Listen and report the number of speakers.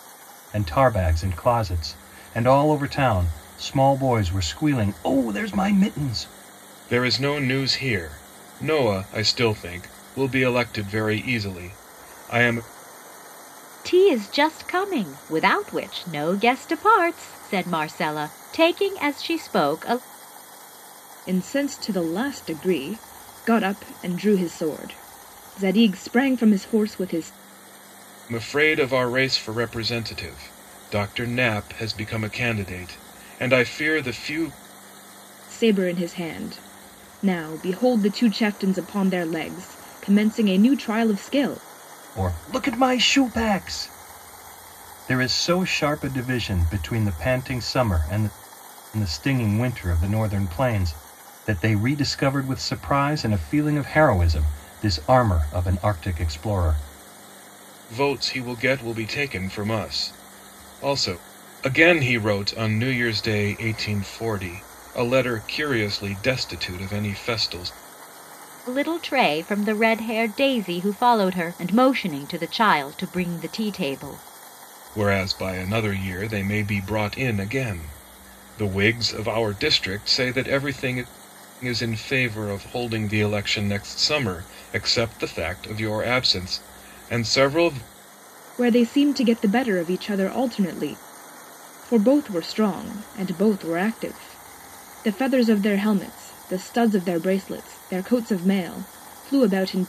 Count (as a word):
four